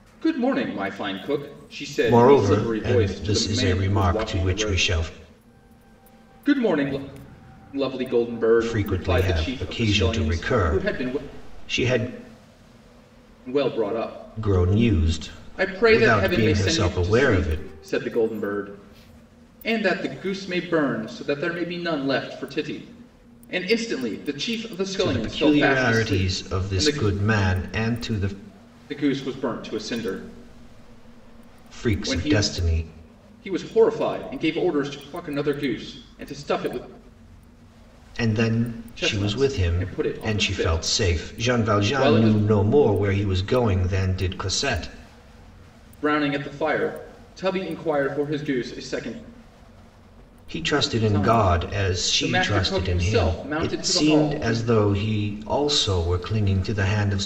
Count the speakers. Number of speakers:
2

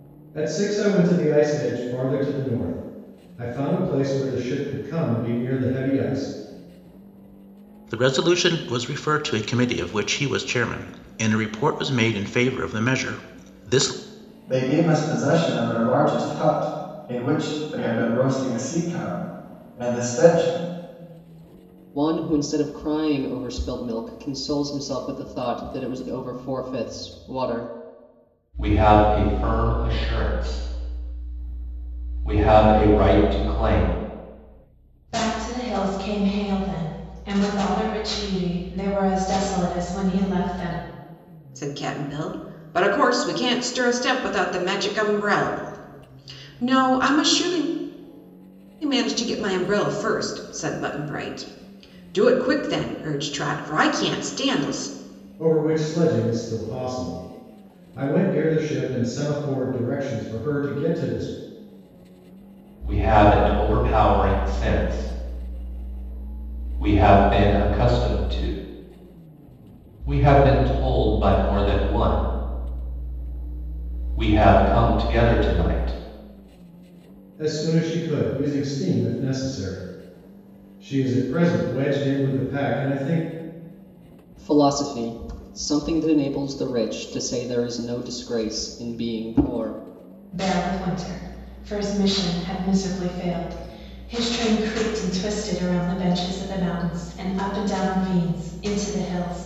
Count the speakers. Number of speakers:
7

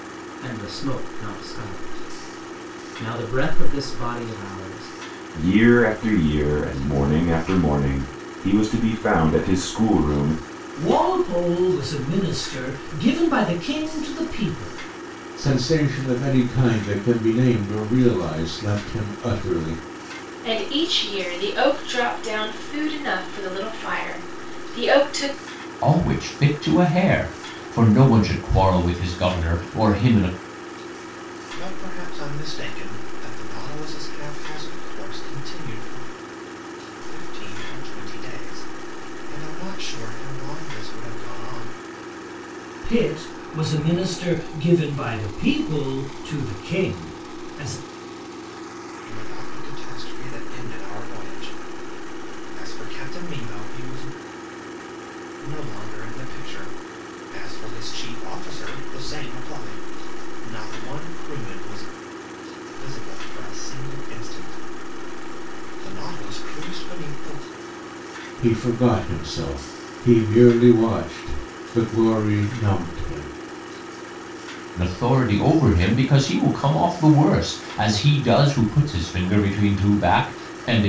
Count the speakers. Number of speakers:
7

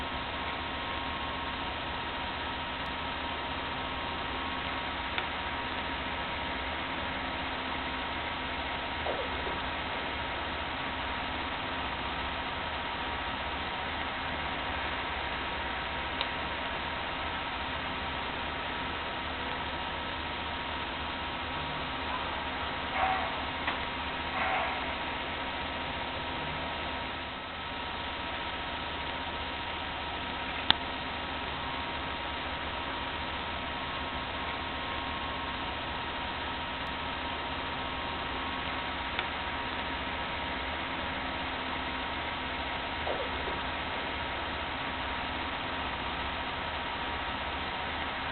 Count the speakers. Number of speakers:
0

